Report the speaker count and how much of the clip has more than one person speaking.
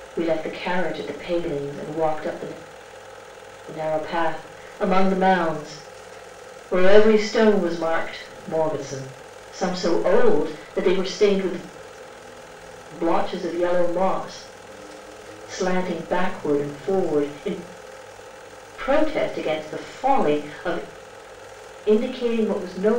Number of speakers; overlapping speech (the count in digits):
1, no overlap